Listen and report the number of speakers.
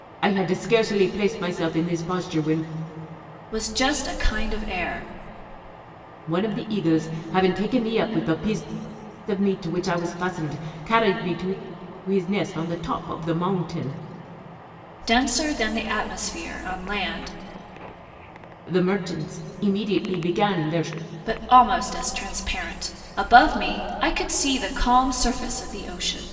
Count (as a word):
two